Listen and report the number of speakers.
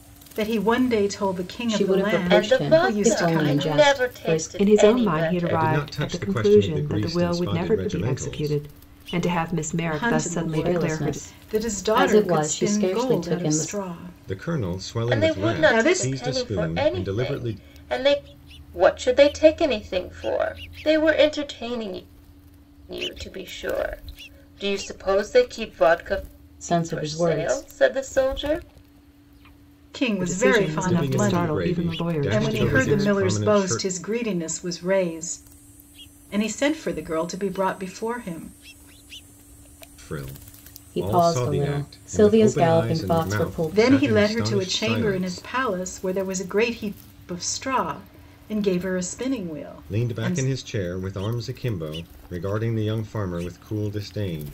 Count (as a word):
five